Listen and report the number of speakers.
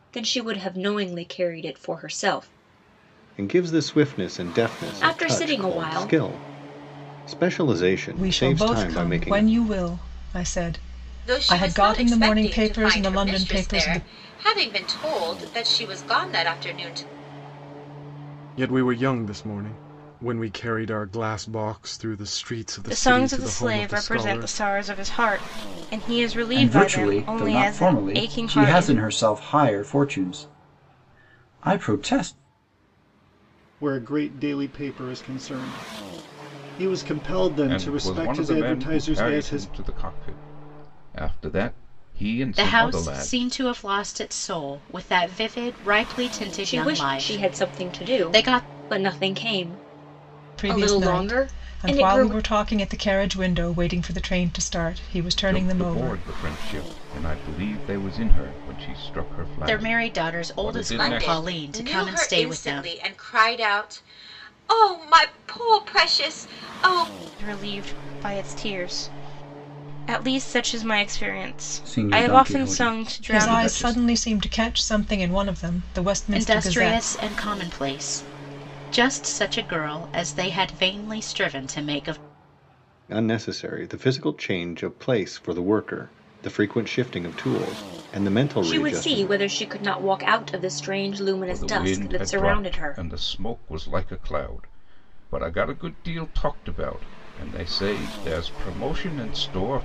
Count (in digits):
10